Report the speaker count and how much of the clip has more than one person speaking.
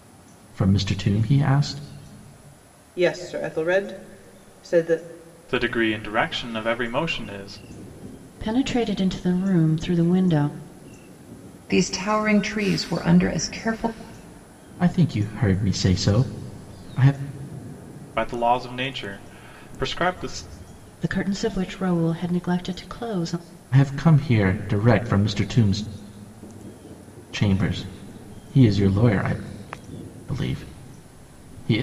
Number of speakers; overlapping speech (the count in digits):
5, no overlap